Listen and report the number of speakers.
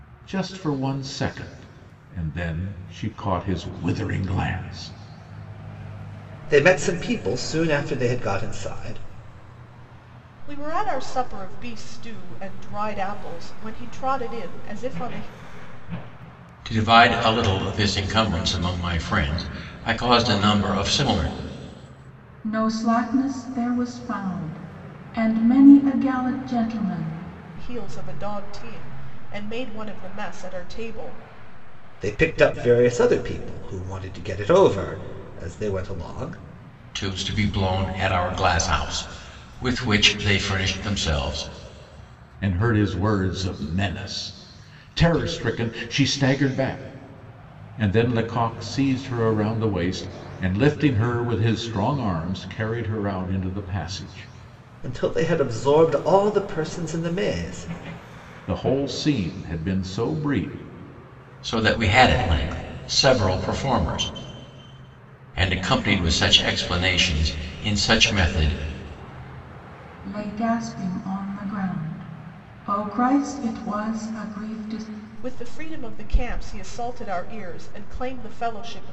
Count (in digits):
5